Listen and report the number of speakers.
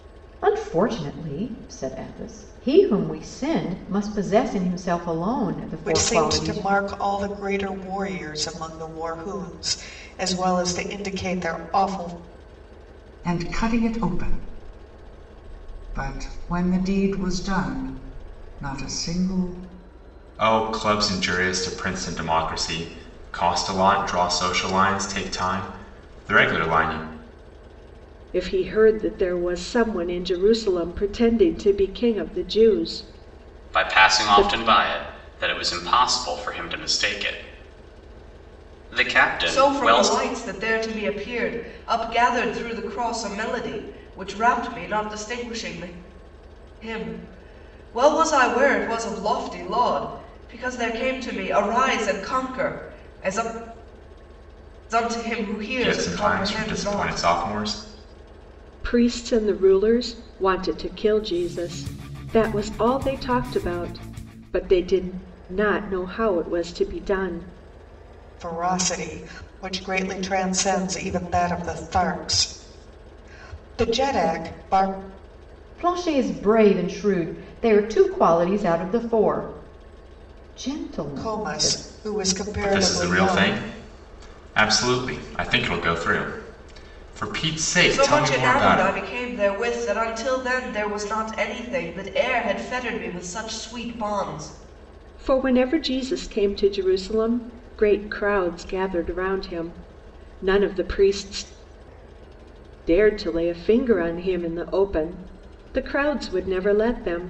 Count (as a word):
seven